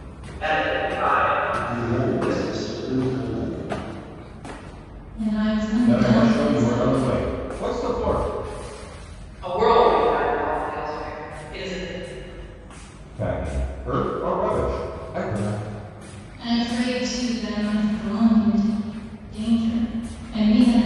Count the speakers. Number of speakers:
five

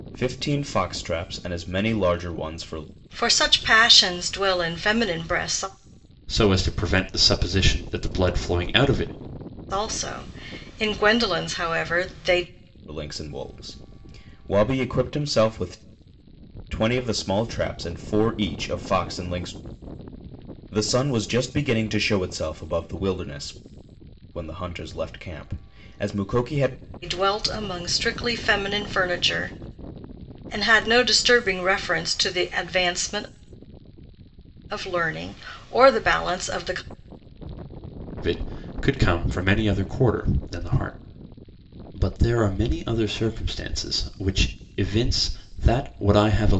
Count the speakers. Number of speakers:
three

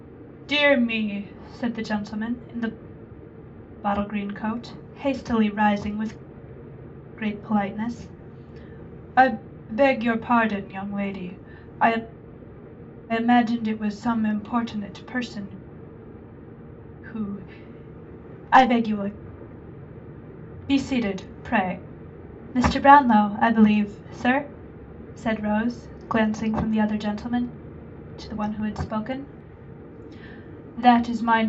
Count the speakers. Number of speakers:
one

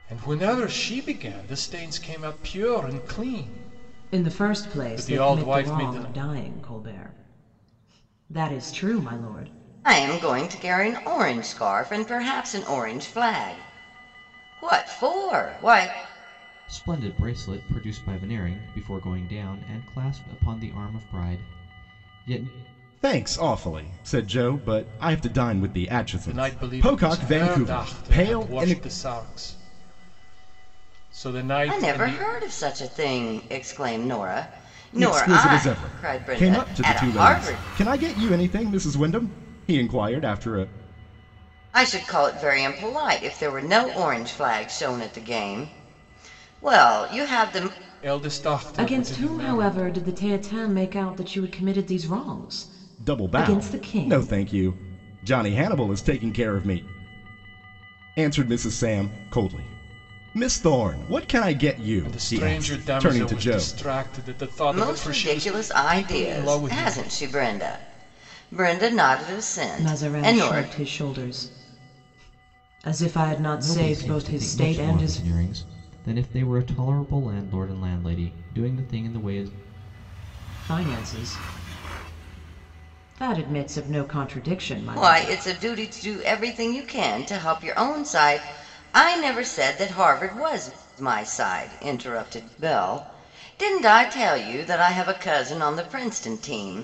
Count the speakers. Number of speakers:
five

